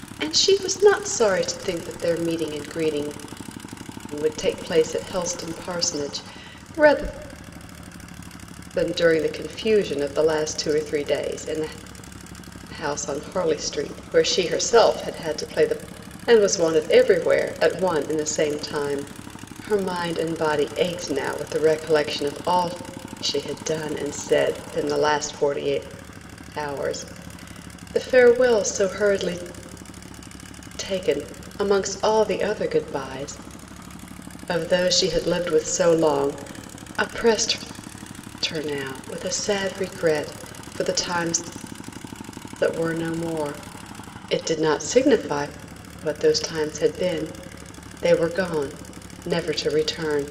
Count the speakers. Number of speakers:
1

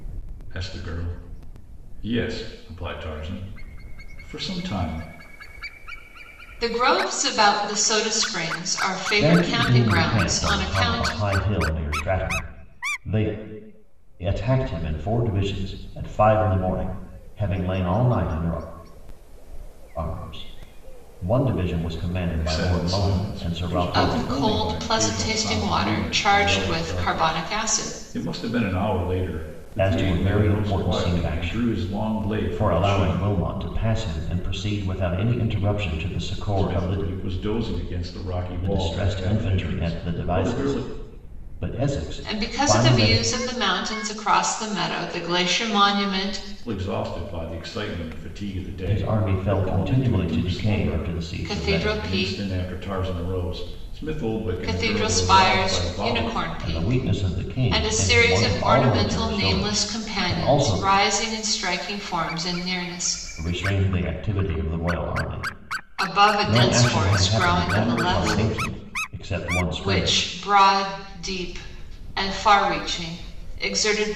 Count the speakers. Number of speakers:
3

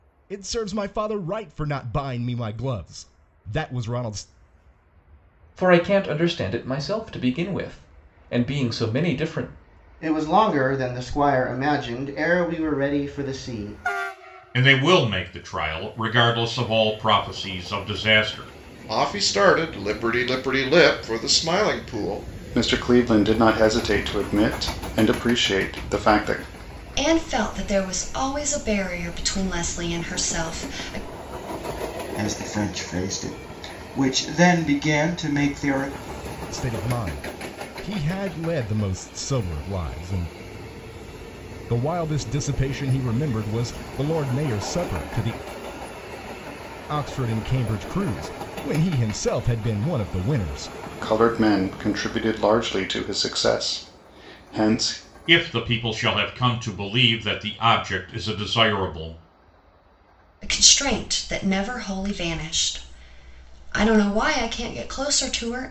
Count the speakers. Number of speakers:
8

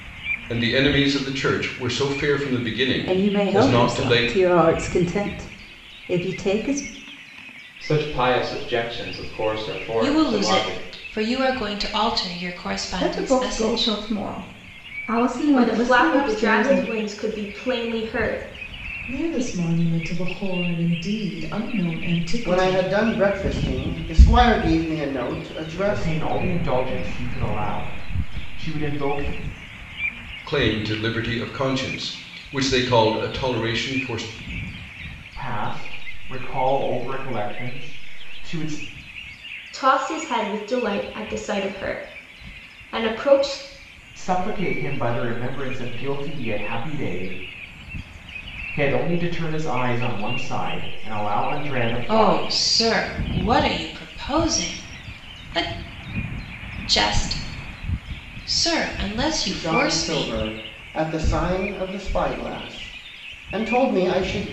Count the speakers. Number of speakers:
9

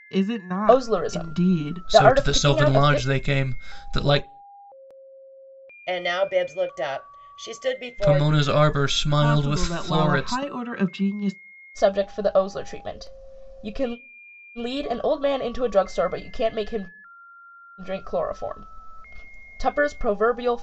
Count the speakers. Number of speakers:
4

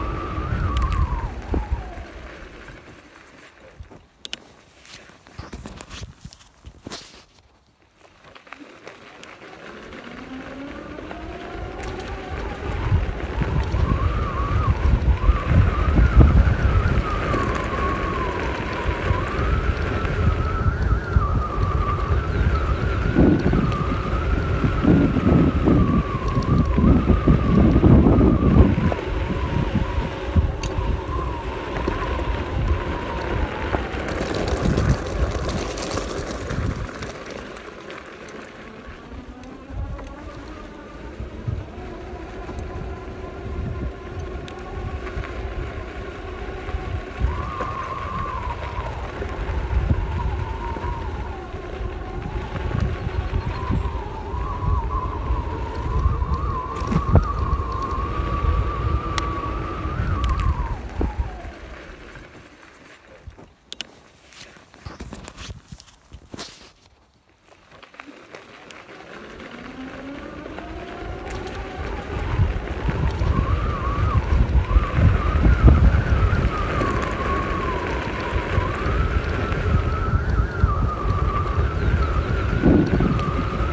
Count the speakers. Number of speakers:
0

